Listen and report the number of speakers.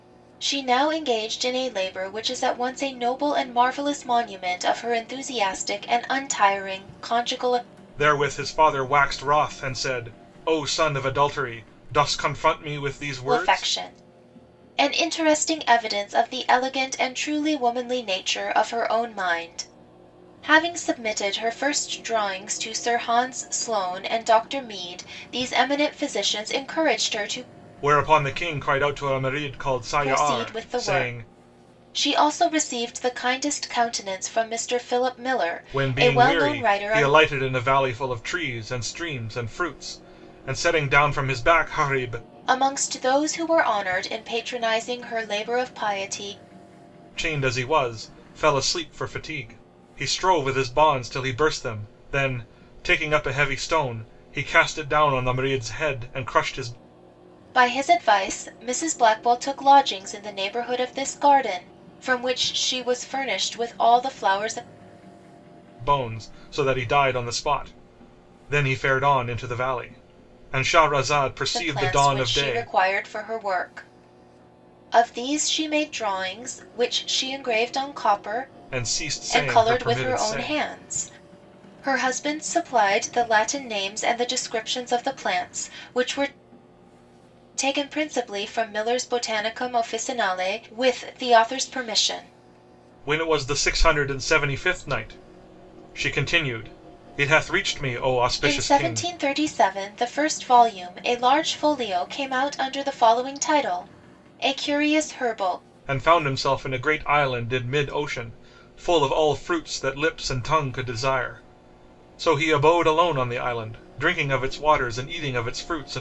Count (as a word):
two